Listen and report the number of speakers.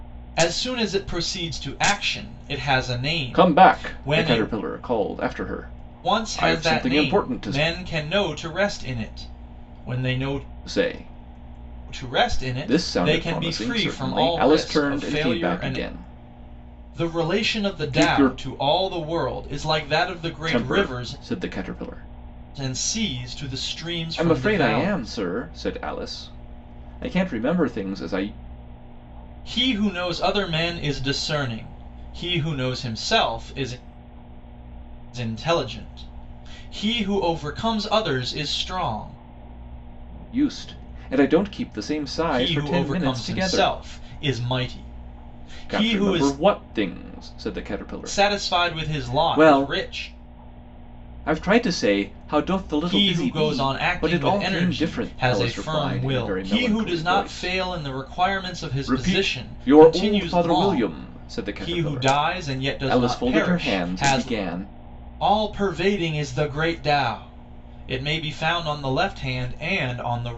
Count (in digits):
2